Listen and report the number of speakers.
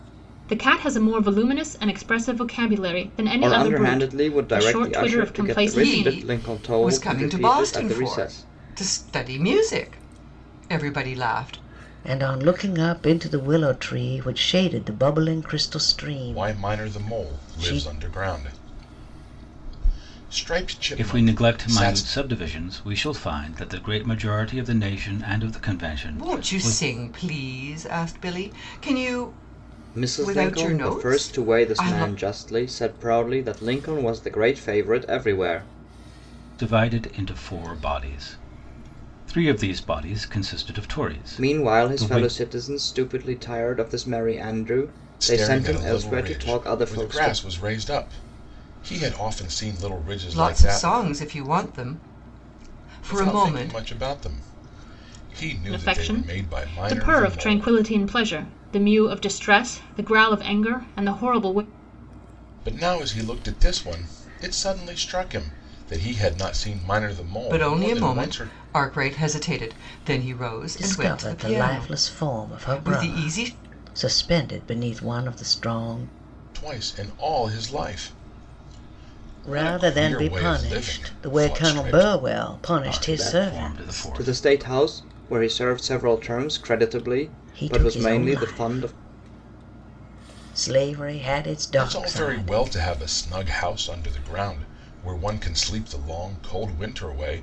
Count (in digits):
6